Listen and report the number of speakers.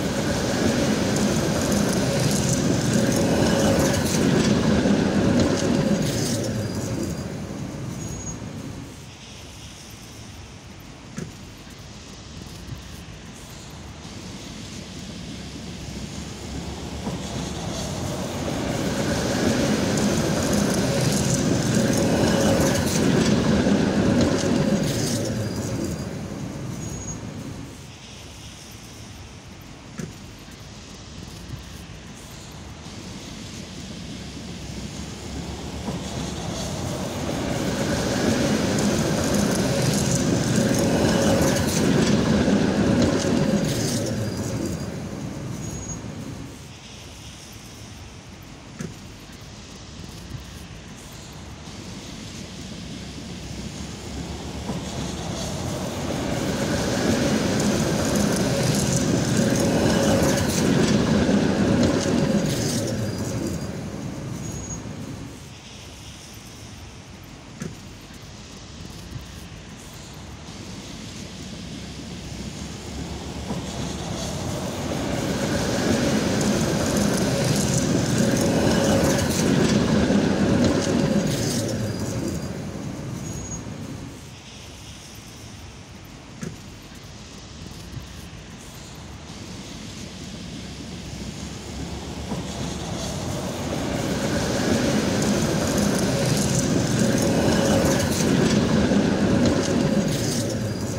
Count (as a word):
zero